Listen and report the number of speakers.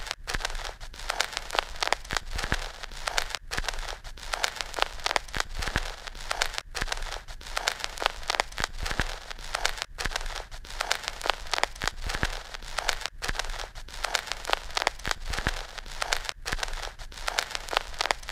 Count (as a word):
zero